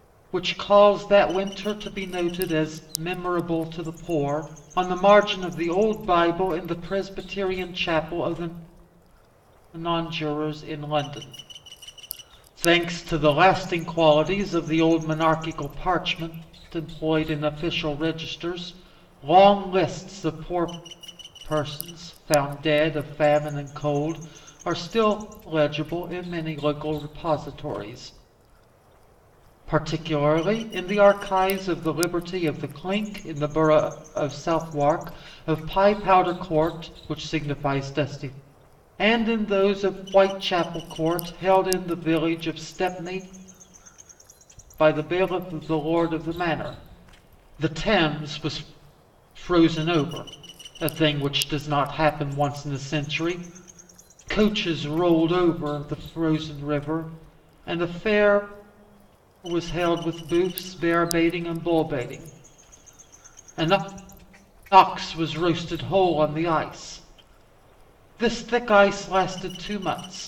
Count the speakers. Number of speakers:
1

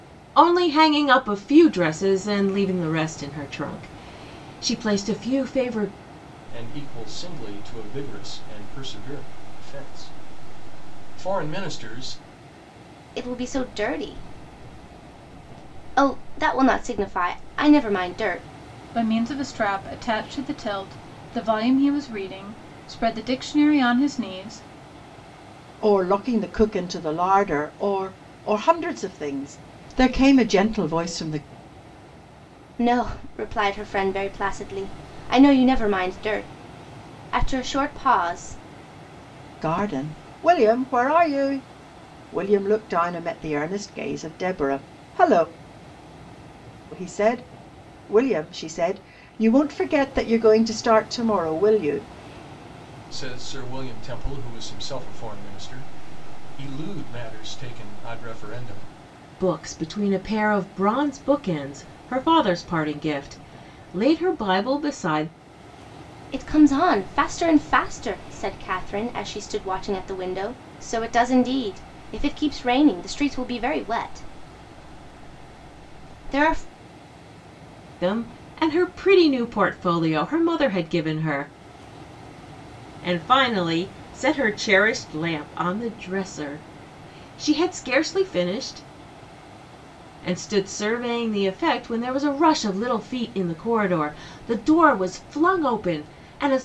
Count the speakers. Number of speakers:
5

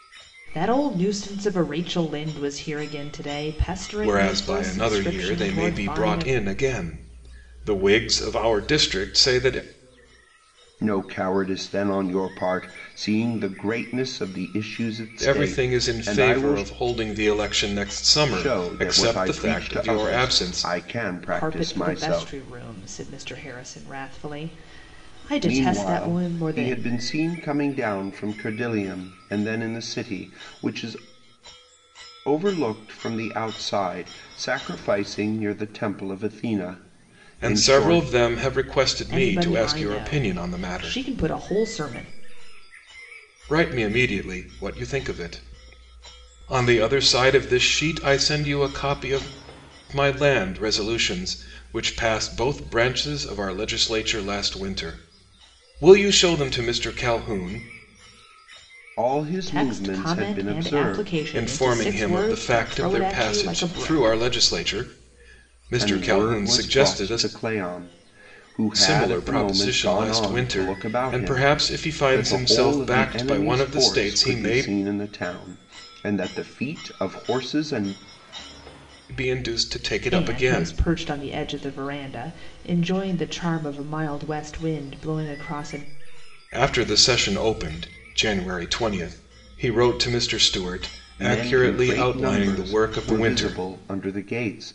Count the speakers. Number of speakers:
3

